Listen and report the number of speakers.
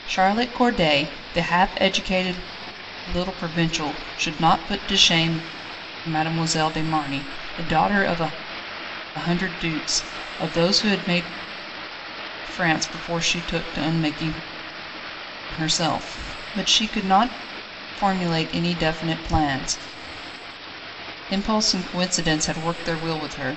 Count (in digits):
1